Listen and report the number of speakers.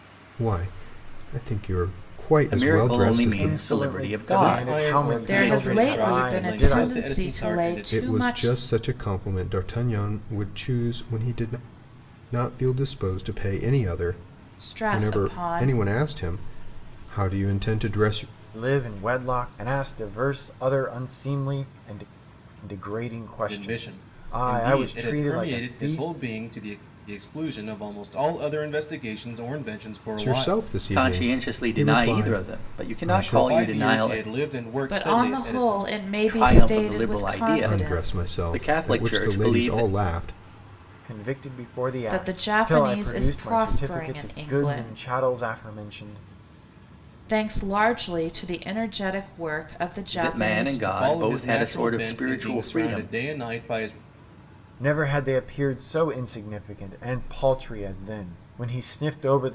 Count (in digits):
5